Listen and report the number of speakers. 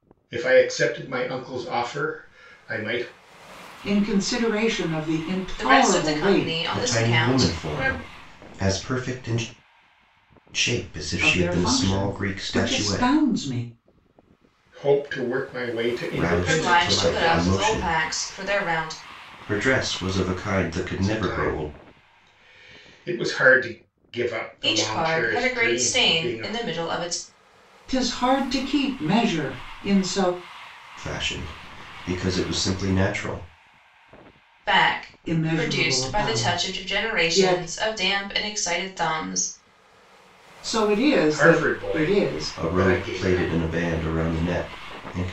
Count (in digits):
4